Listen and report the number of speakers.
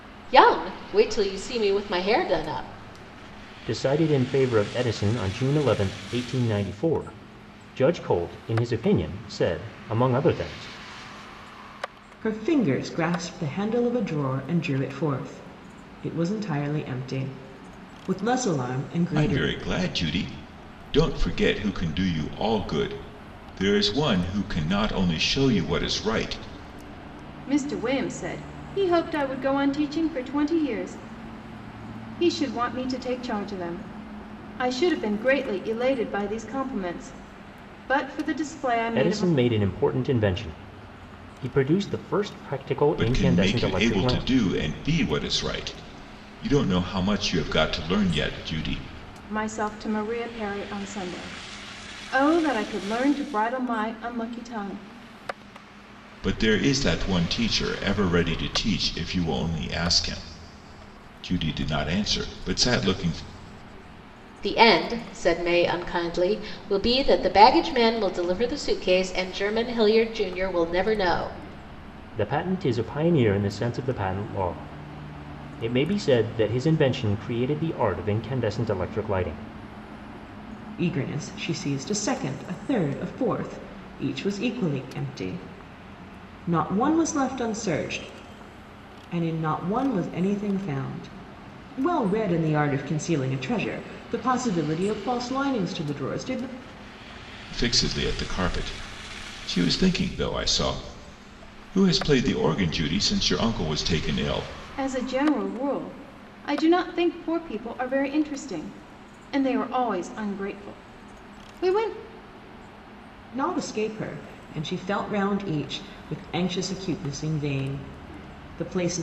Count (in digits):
5